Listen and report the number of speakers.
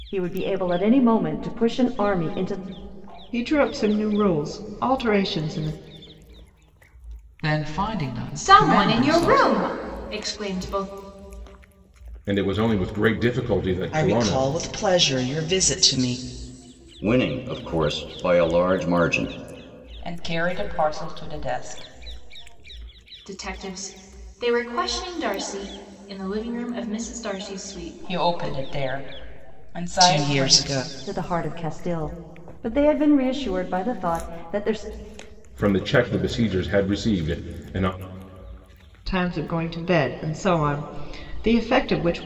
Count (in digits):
8